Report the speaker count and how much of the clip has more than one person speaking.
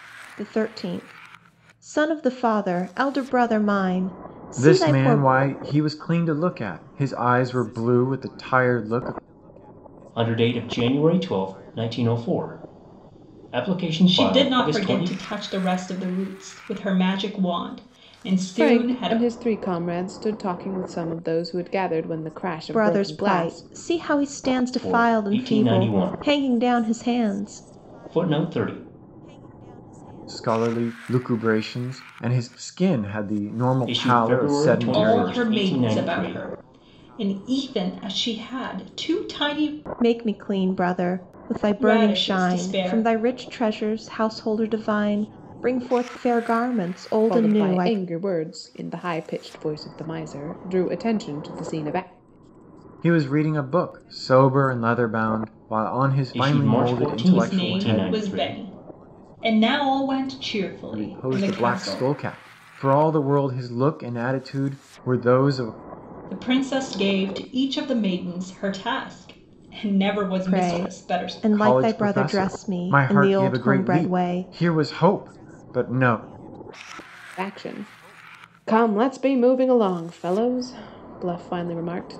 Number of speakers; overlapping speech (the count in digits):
5, about 23%